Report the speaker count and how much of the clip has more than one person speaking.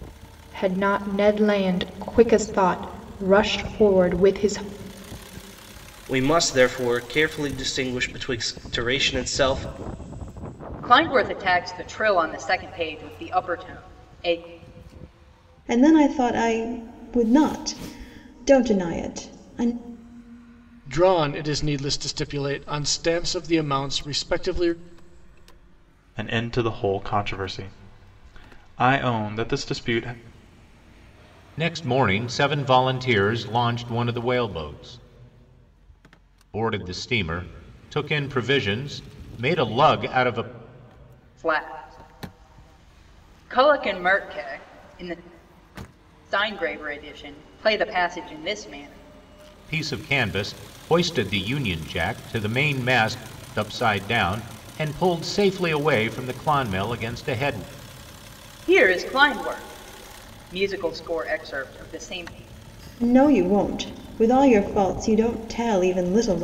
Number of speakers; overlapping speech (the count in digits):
7, no overlap